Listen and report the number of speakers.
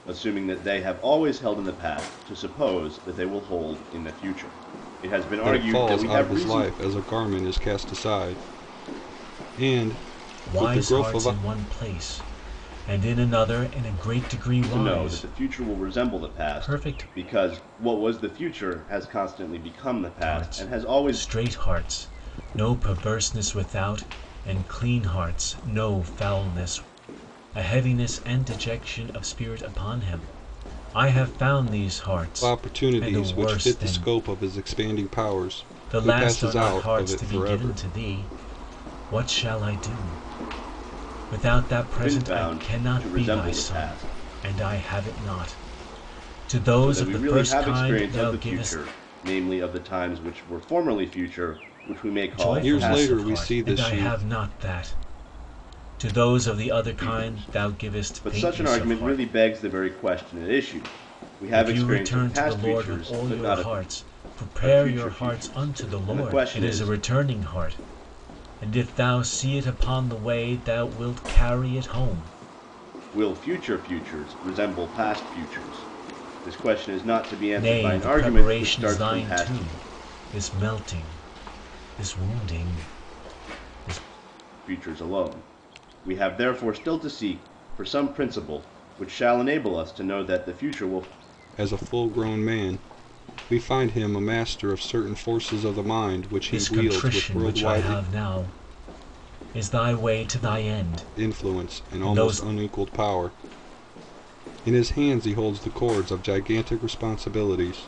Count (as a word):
three